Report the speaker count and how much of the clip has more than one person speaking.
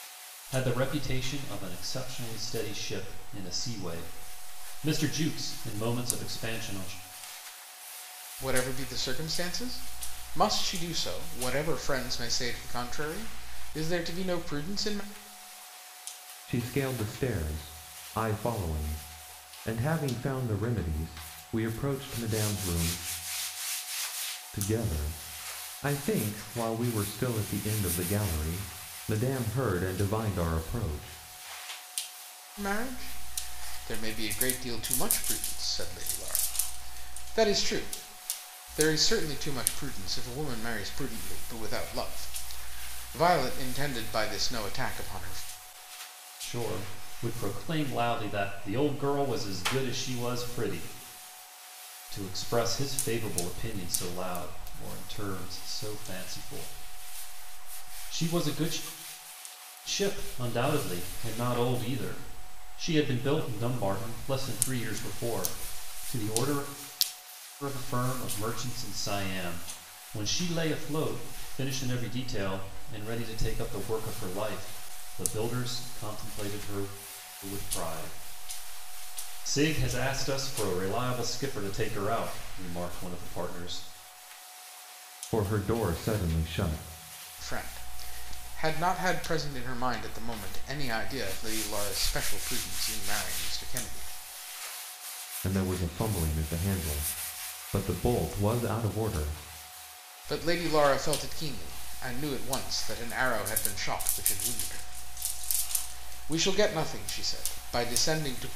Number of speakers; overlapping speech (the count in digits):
3, no overlap